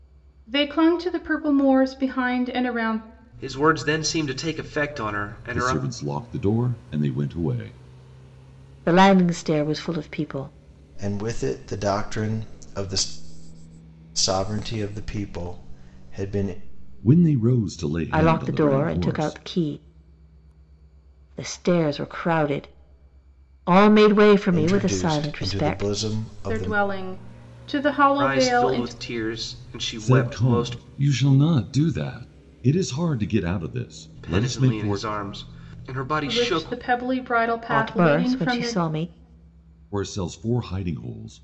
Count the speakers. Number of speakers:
5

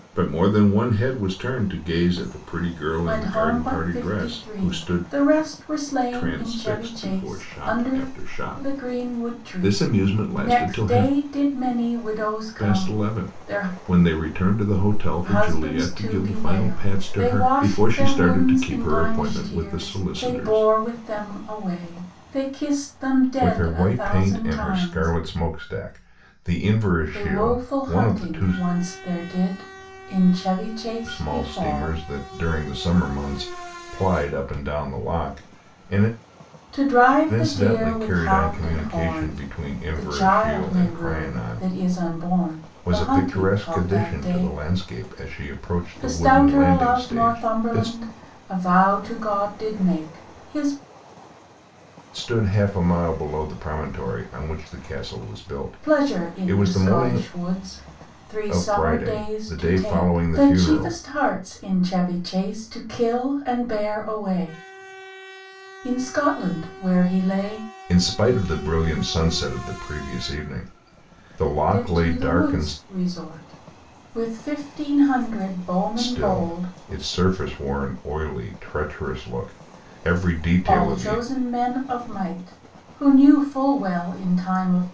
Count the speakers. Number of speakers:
2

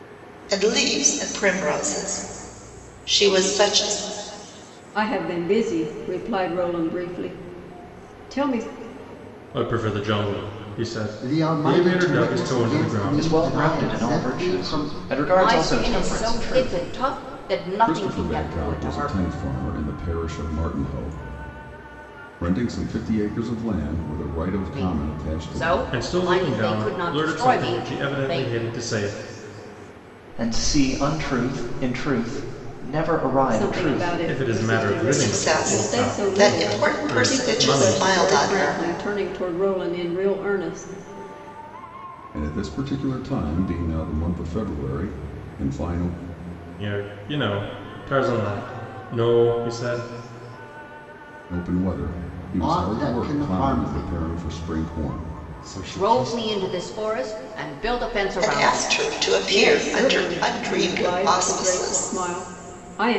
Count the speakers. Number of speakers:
7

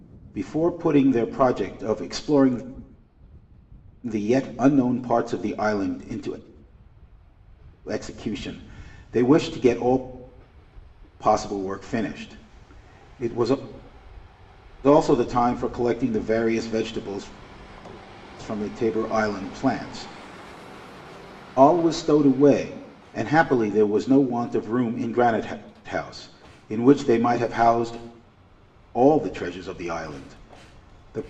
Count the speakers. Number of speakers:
1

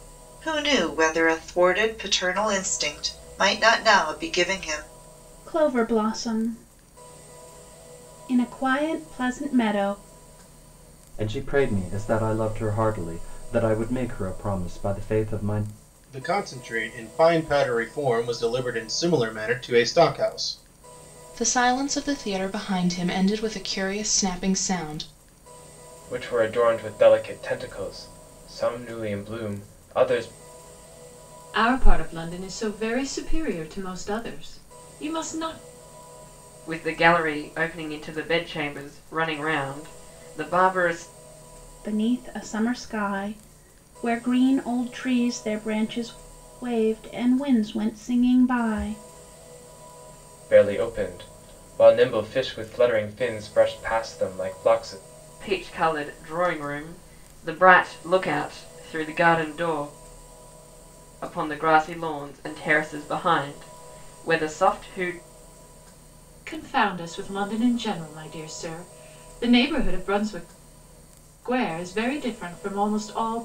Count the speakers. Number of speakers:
8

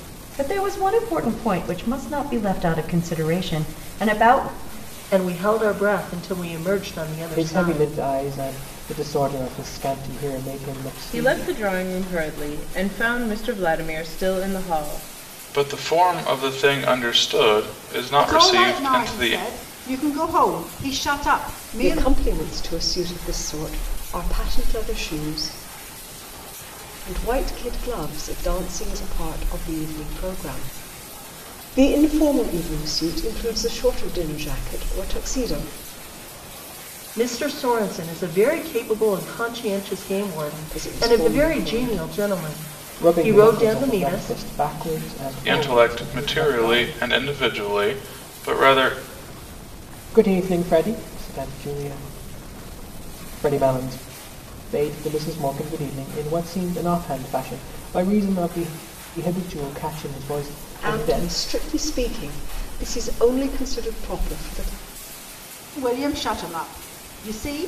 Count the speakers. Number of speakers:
7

